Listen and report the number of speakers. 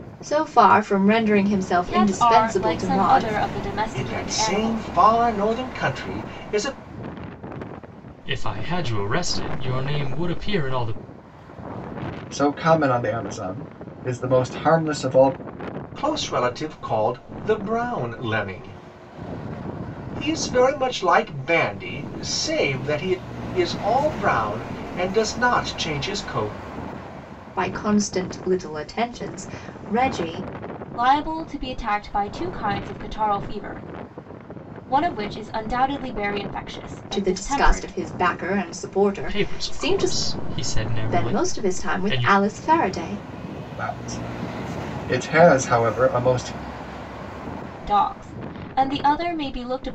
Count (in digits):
5